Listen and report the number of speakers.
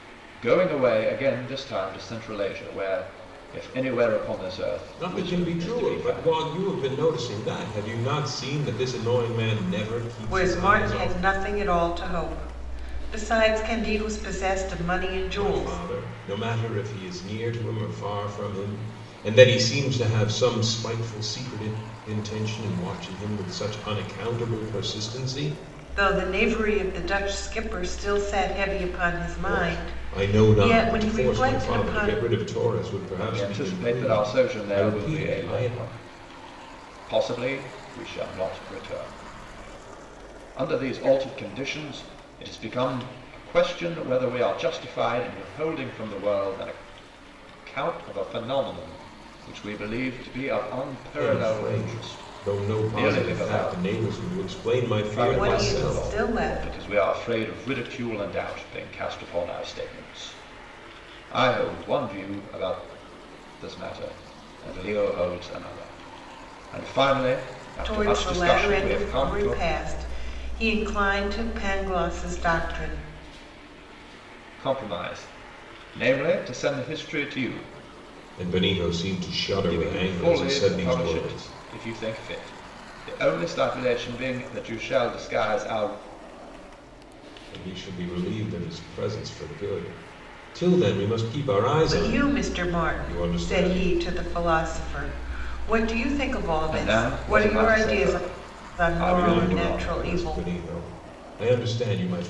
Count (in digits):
3